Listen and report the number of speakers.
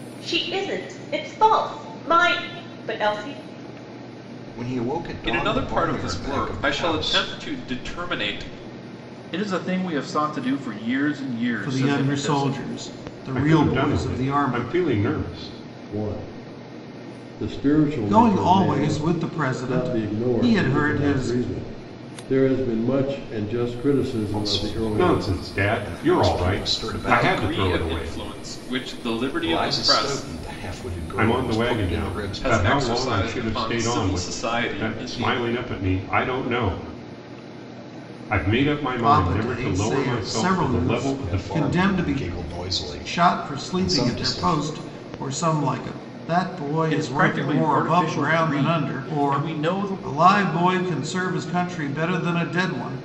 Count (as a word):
seven